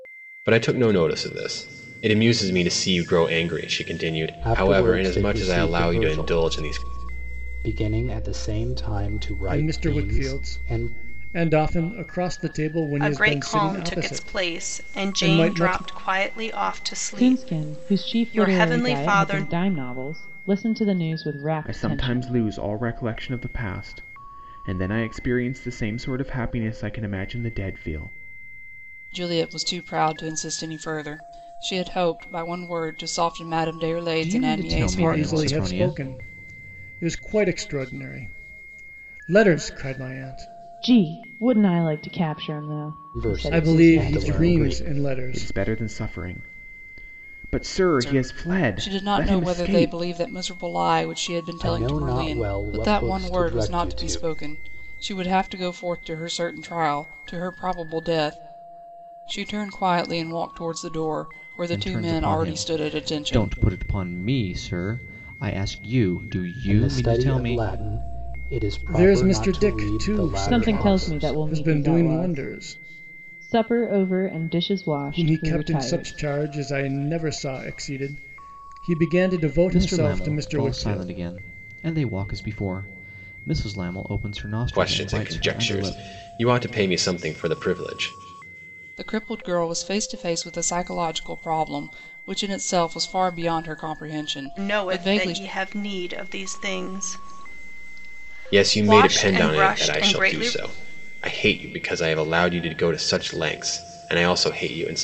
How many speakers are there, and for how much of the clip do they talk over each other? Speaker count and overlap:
8, about 31%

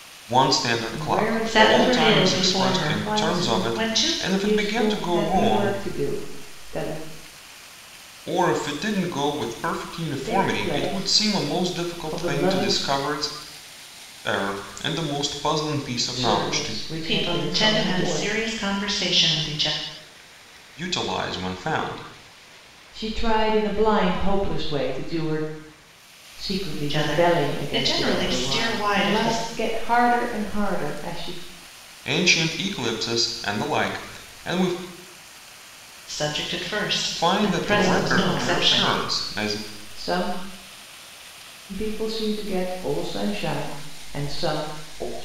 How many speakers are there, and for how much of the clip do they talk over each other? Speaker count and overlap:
3, about 32%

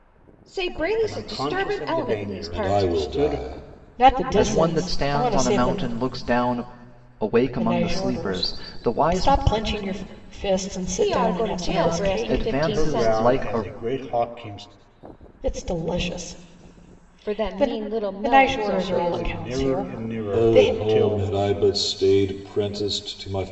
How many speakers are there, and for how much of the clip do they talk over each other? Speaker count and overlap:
5, about 51%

